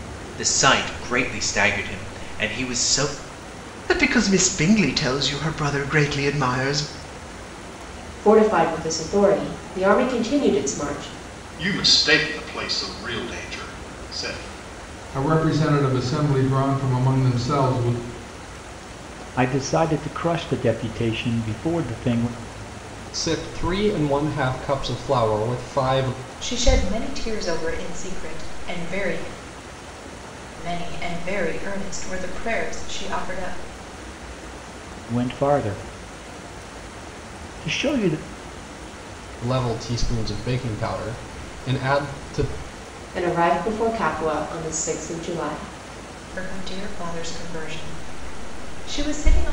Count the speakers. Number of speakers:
8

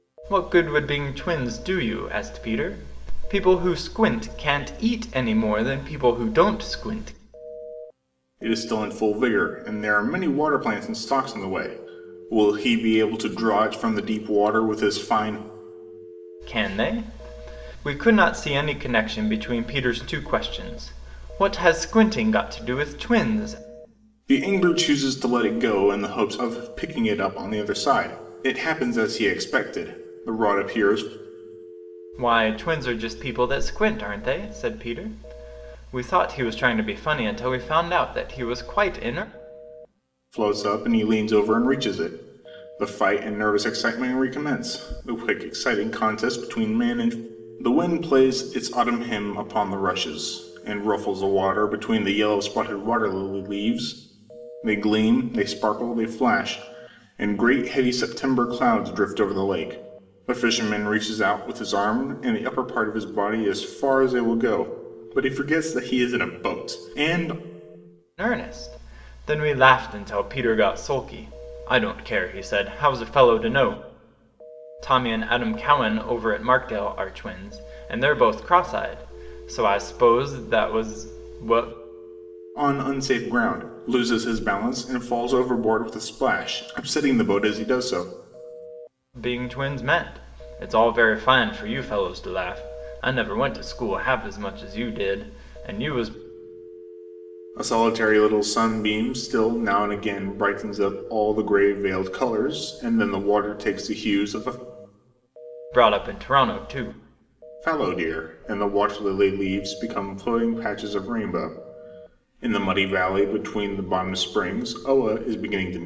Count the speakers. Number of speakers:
2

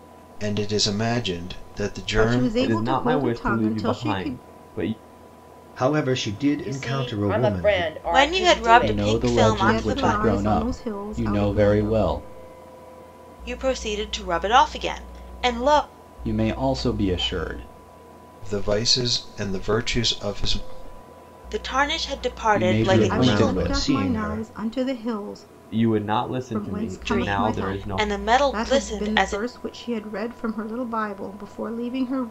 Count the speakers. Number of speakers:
7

